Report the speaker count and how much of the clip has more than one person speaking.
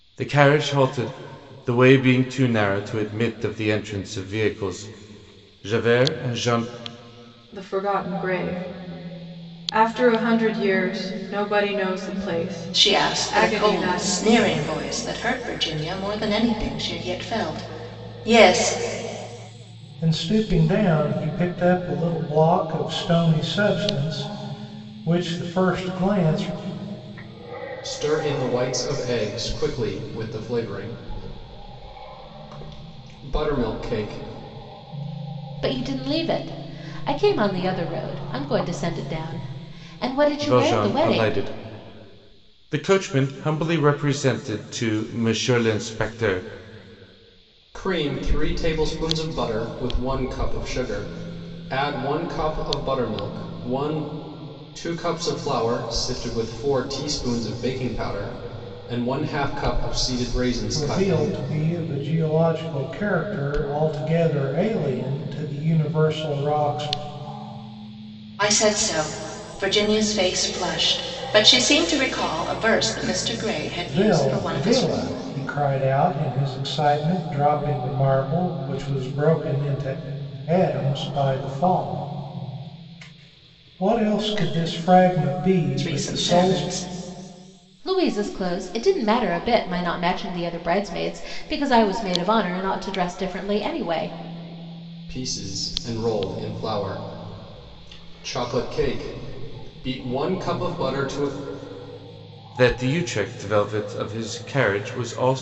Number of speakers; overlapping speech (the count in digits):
6, about 4%